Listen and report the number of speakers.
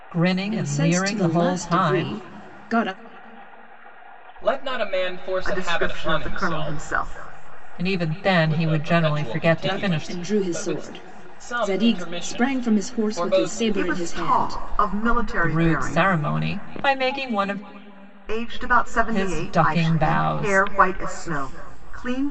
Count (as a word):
four